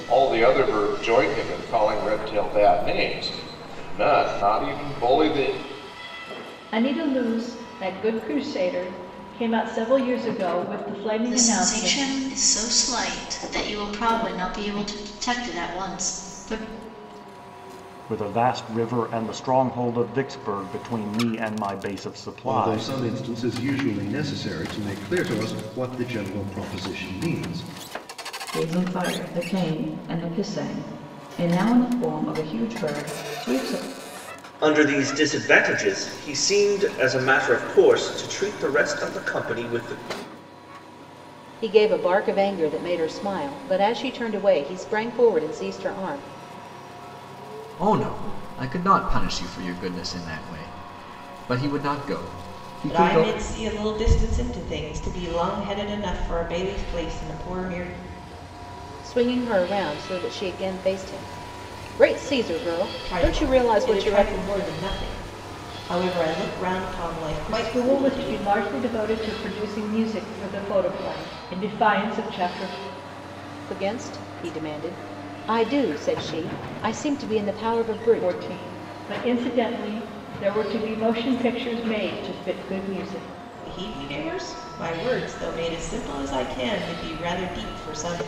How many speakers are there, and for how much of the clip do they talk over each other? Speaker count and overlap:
10, about 5%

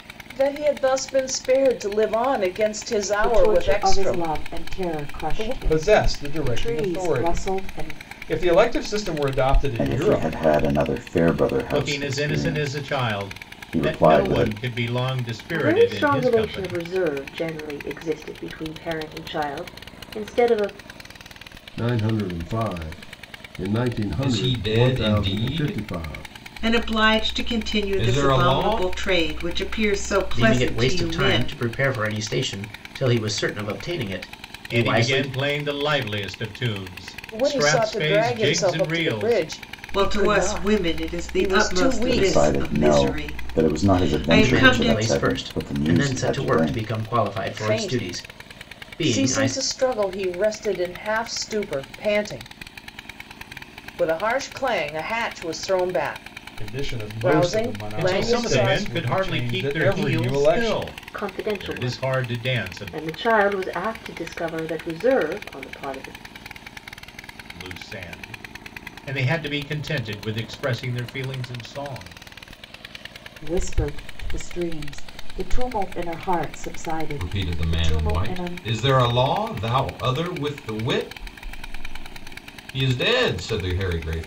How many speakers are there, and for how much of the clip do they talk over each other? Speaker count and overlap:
10, about 42%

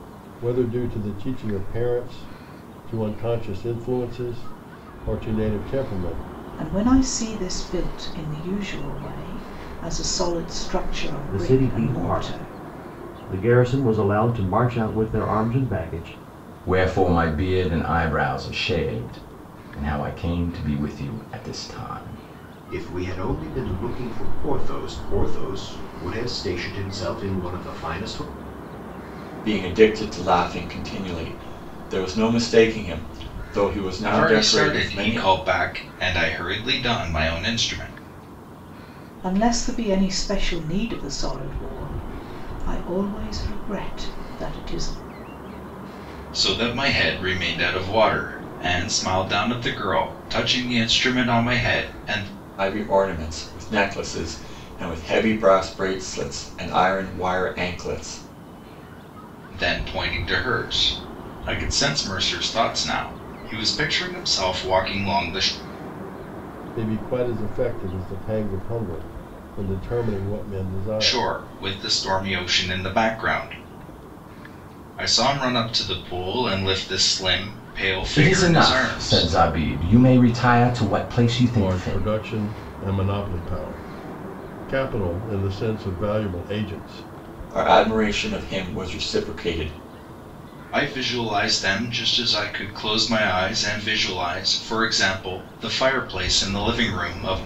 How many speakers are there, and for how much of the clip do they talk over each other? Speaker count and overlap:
7, about 5%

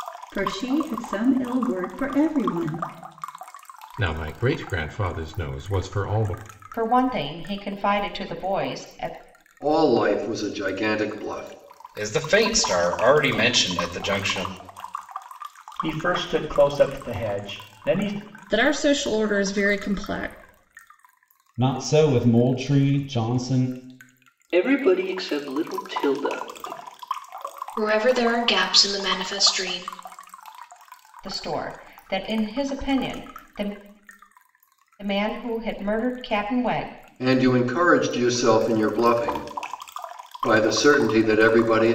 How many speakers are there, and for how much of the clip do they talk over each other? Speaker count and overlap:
10, no overlap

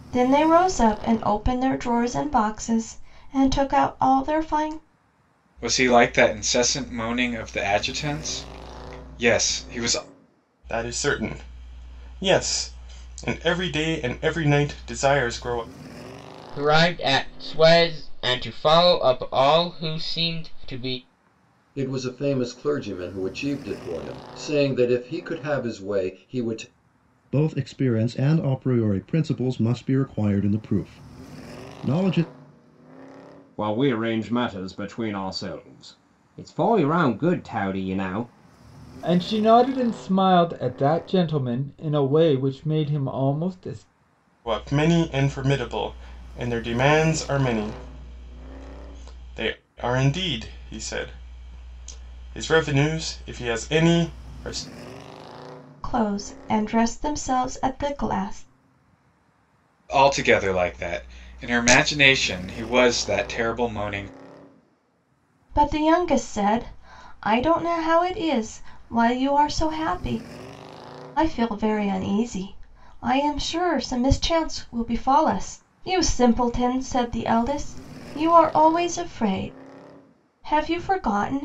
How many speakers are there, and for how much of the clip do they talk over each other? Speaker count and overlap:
8, no overlap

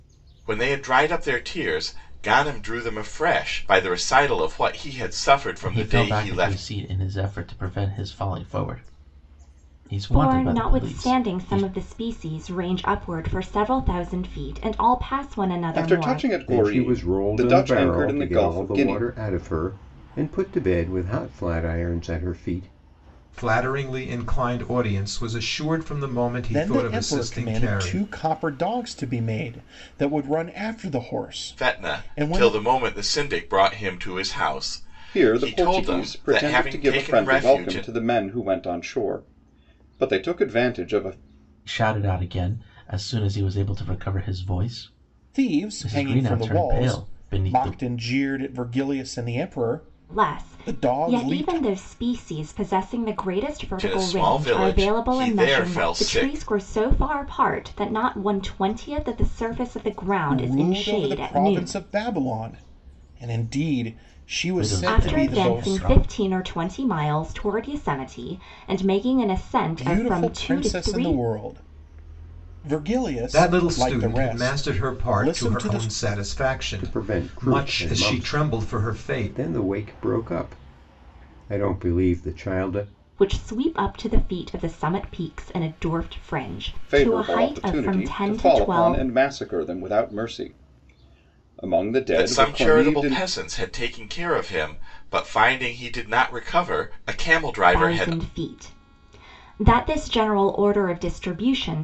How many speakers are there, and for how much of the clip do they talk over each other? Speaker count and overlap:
7, about 32%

